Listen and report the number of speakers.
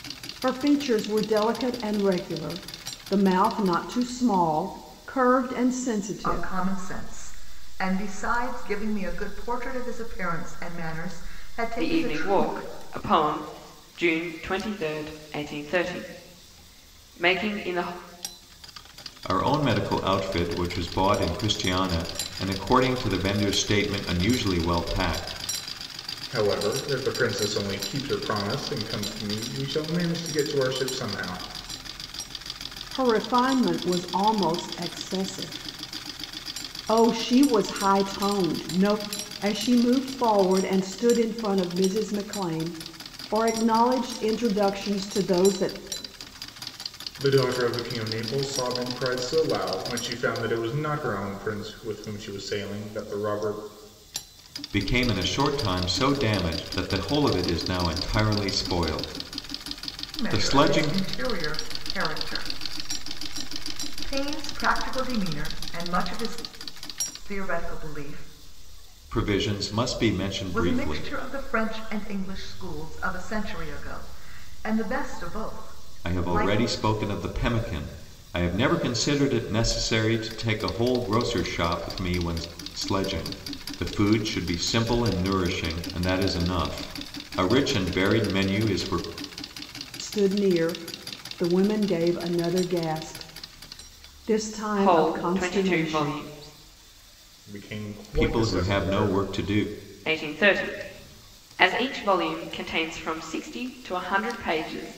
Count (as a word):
five